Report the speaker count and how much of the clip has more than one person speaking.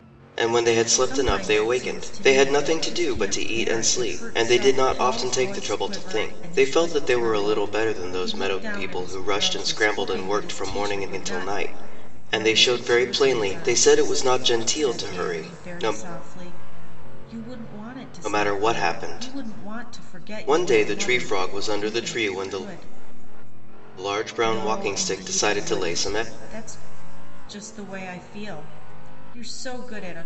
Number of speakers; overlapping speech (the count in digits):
2, about 59%